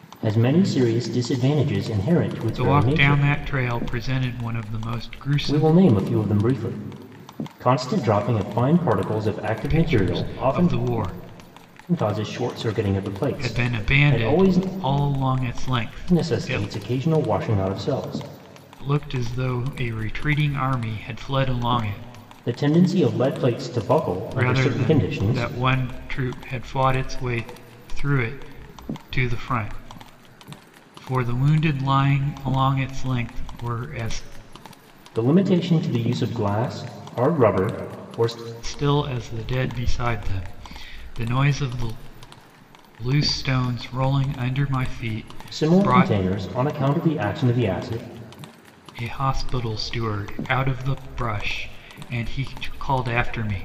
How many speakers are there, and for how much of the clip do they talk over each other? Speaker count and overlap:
two, about 11%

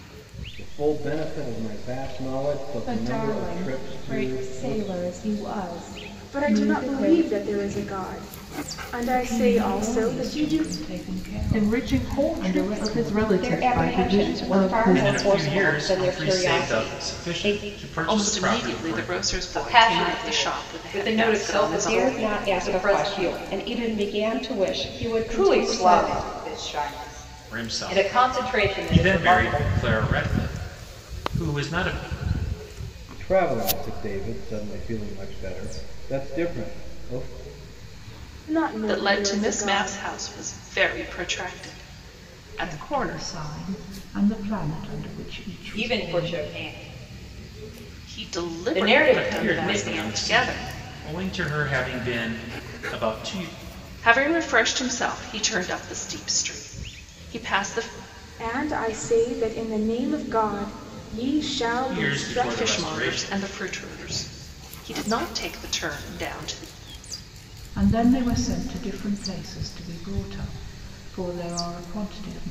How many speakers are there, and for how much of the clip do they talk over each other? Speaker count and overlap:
nine, about 36%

